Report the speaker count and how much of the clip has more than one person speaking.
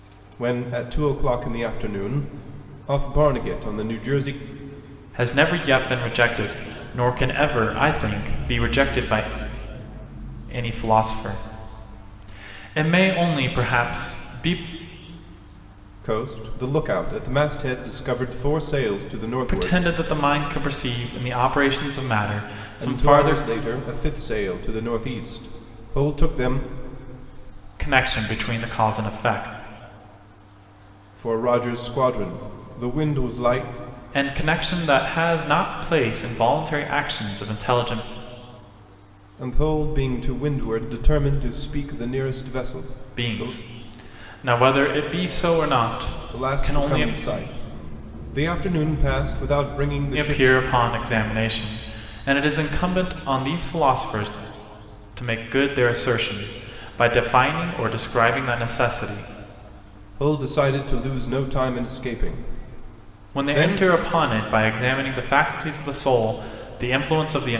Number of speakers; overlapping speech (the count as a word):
two, about 5%